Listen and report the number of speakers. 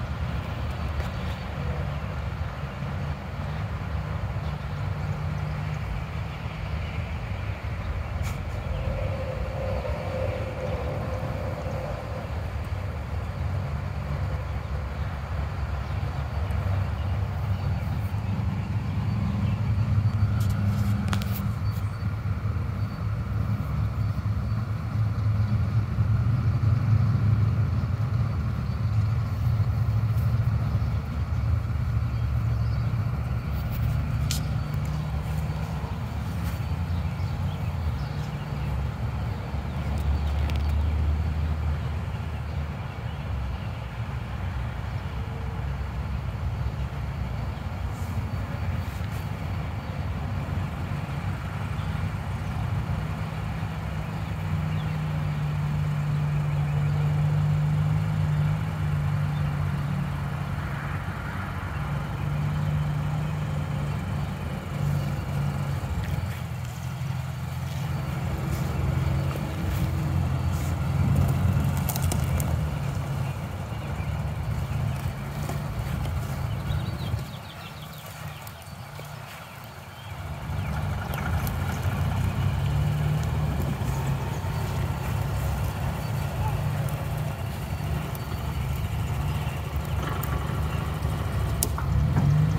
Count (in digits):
0